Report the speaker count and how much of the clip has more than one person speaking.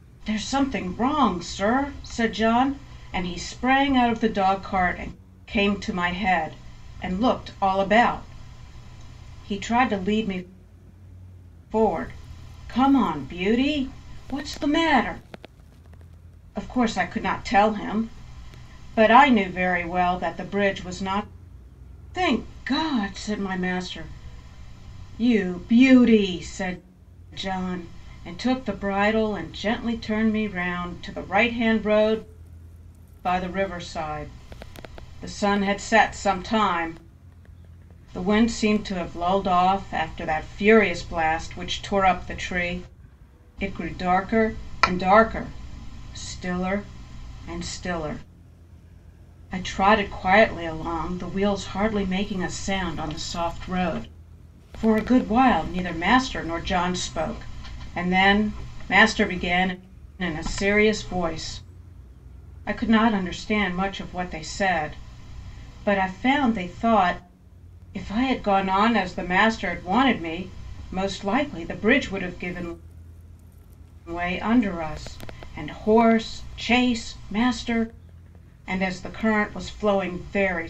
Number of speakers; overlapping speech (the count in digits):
1, no overlap